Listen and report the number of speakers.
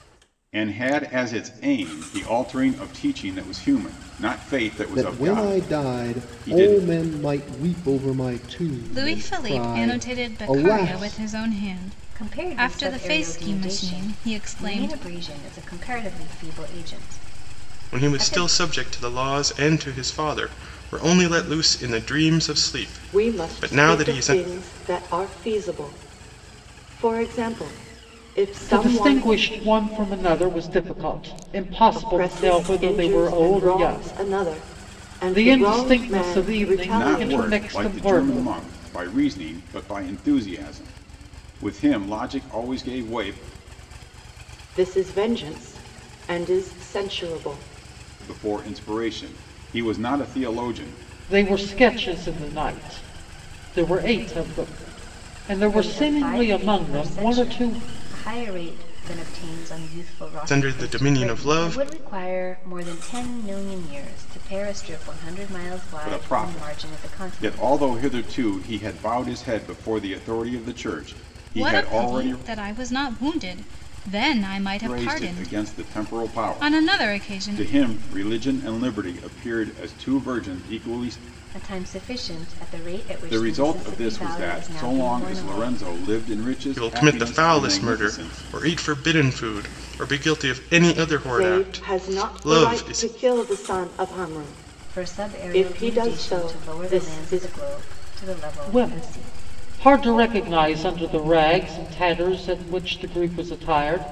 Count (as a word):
seven